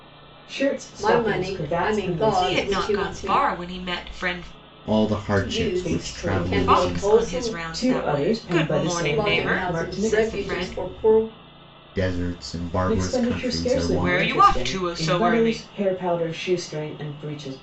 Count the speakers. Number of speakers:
four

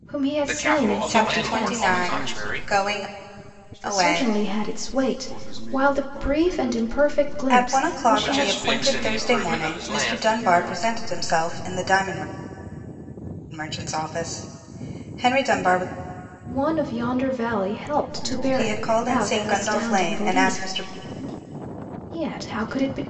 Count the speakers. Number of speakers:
four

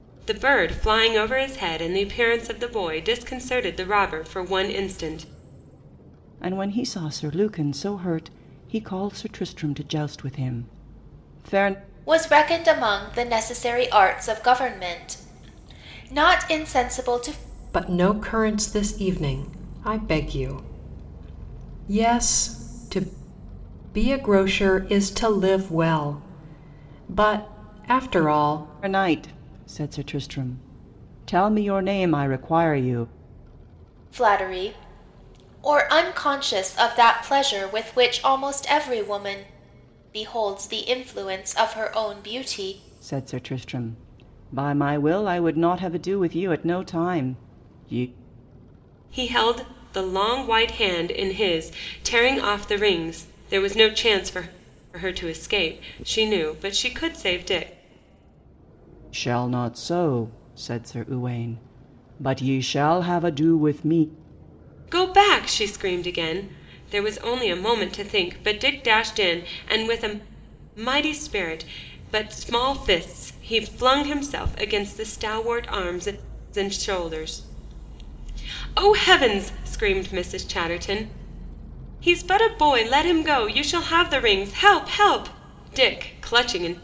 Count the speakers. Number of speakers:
four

